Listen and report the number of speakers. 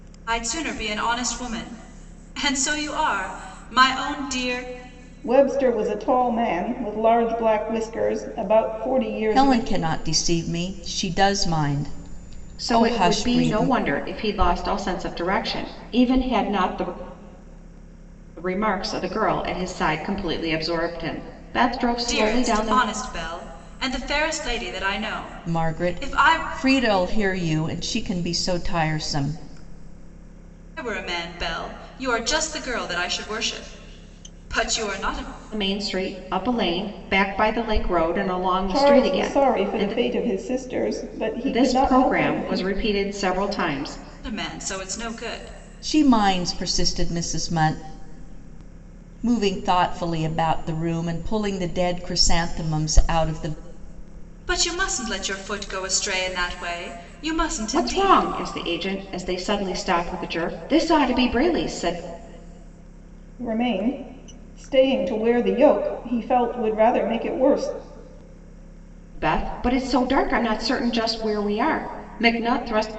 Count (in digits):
4